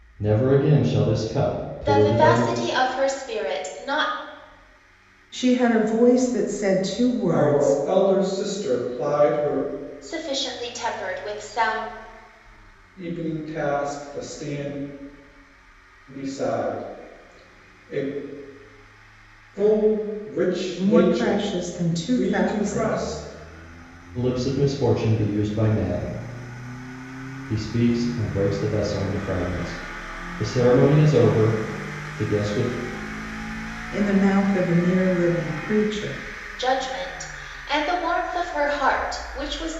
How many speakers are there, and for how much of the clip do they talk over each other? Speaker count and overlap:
4, about 7%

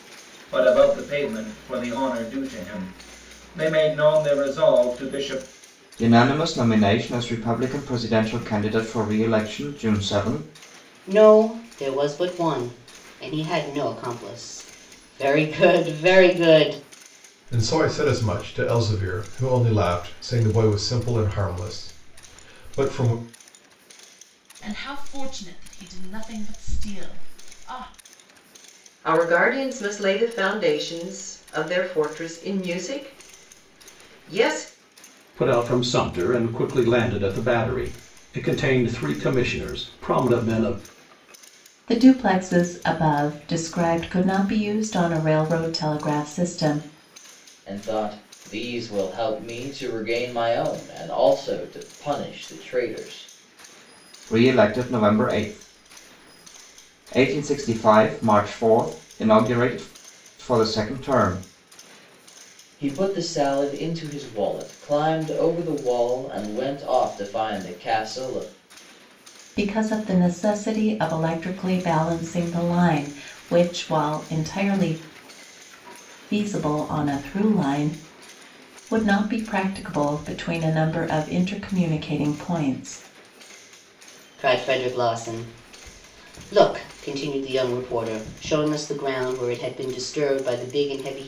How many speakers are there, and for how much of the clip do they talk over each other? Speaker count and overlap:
9, no overlap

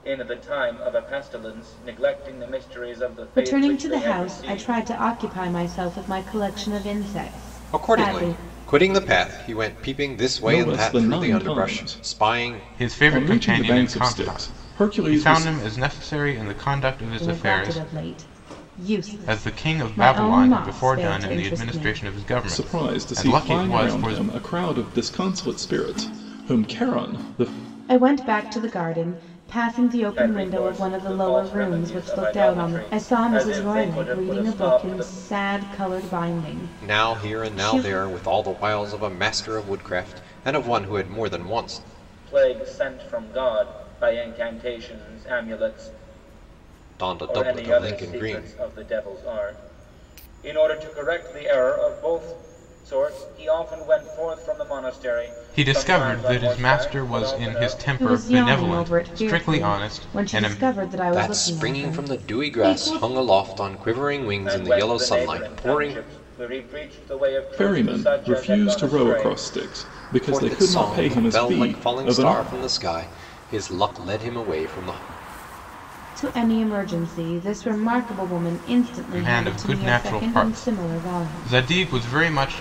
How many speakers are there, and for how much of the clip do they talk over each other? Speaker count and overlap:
5, about 42%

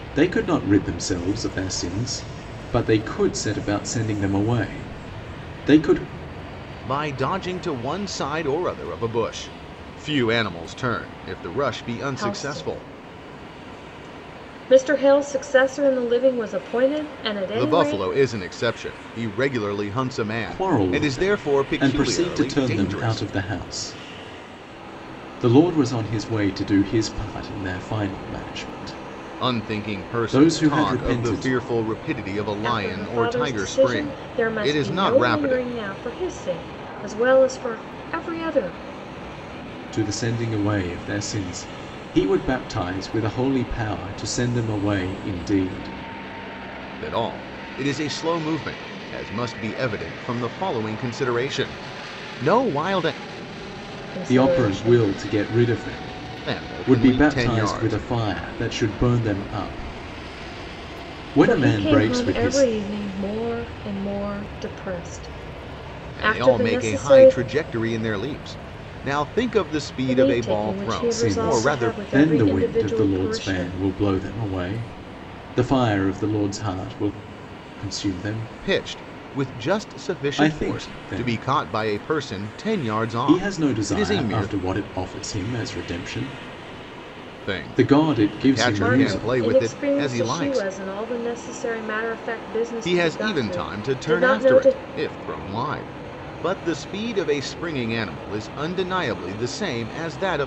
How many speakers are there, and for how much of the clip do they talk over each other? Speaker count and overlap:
3, about 27%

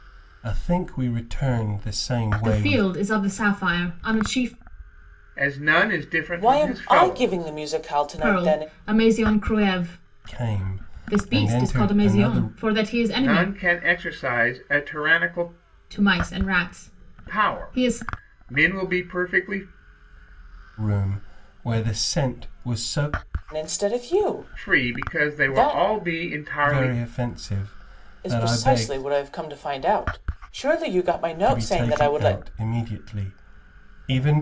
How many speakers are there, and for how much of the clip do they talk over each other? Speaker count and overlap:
4, about 25%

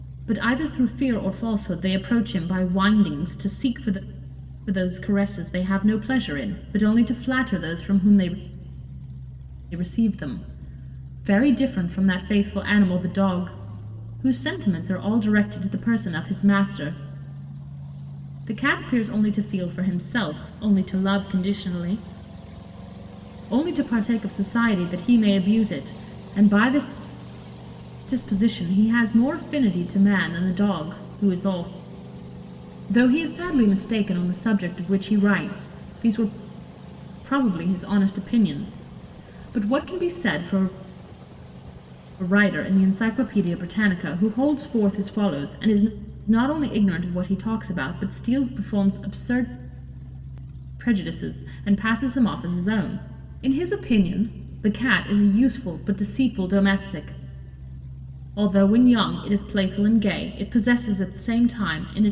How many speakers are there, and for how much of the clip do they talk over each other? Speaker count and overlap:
1, no overlap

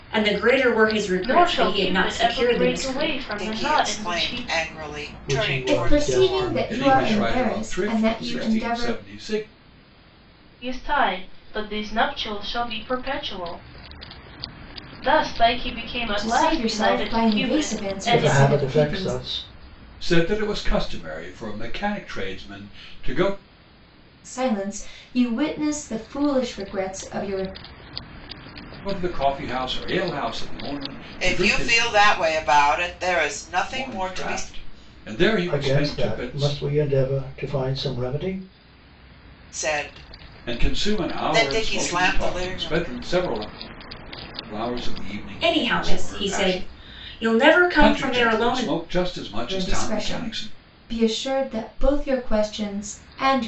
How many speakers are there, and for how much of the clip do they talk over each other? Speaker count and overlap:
6, about 34%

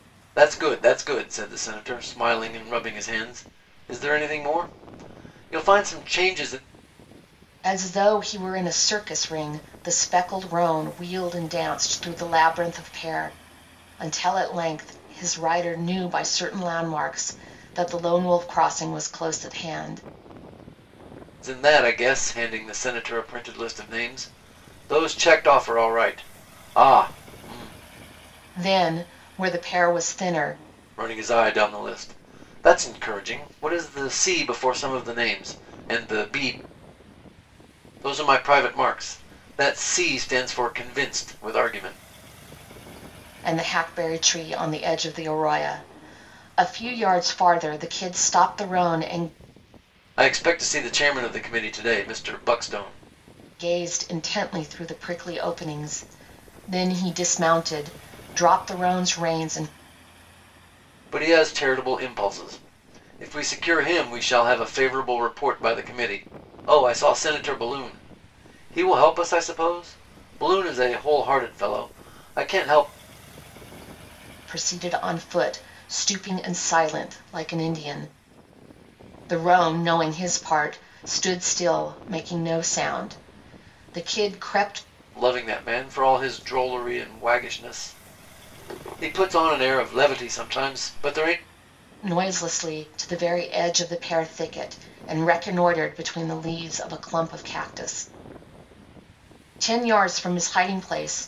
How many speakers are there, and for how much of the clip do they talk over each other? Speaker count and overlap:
2, no overlap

